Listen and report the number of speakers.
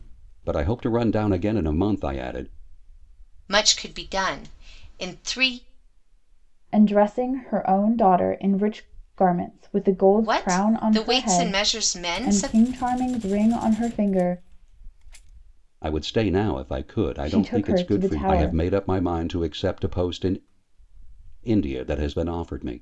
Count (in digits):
3